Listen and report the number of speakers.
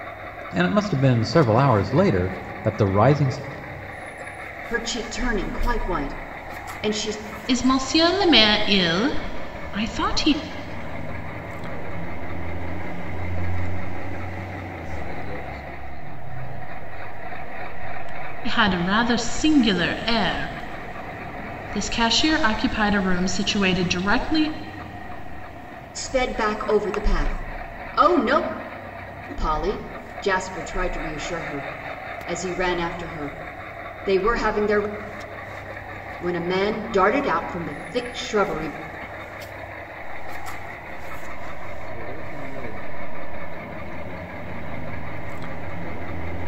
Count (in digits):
4